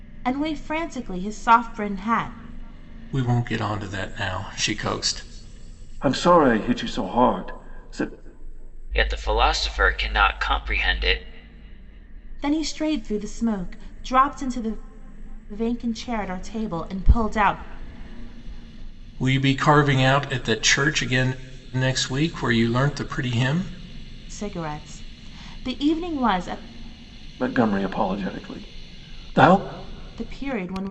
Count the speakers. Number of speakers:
four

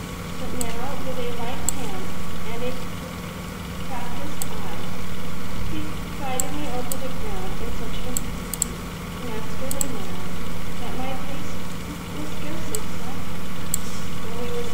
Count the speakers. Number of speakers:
one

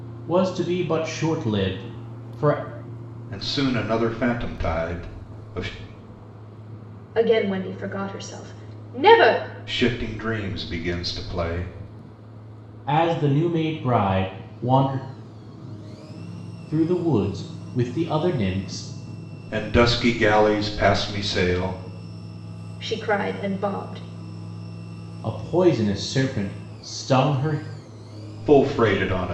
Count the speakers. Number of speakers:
three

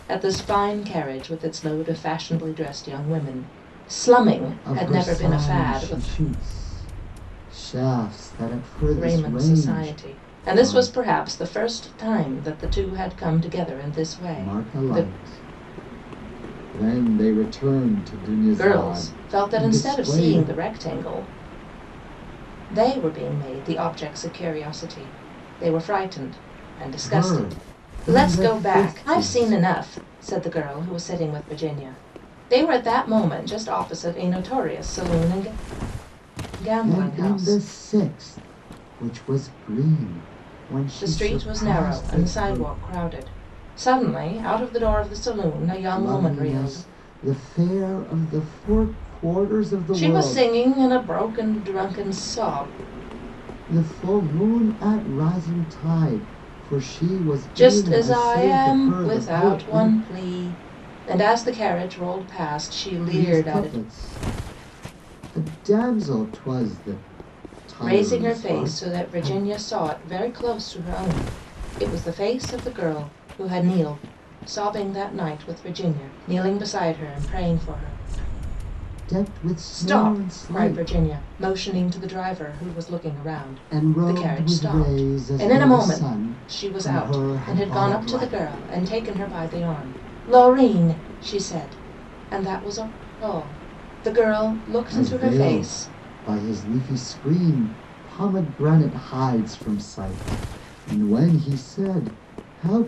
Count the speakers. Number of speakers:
two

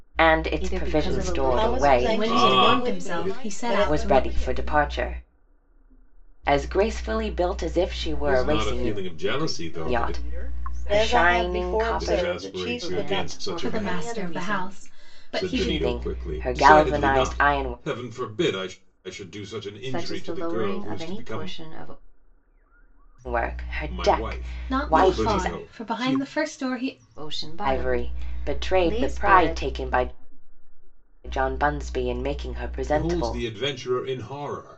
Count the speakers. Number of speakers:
six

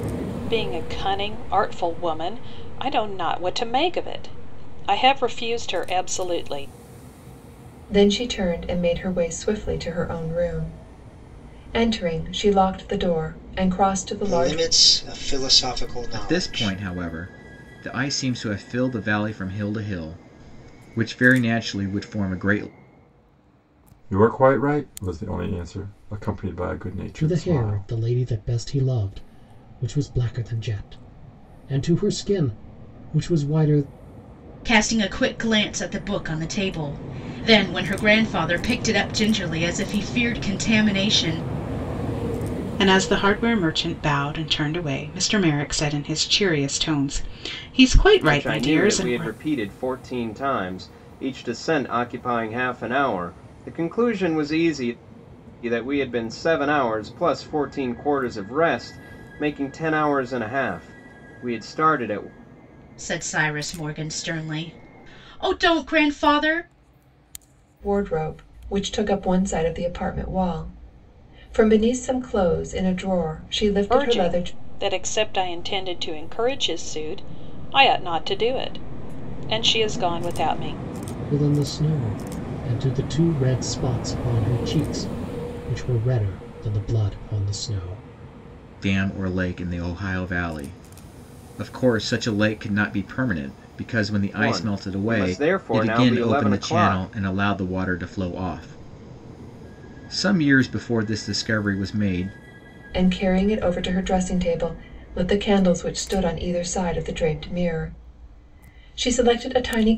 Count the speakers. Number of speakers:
nine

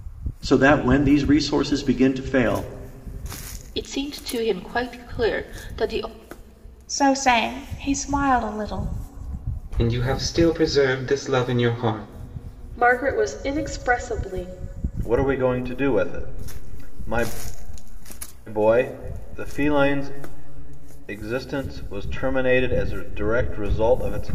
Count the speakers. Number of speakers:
six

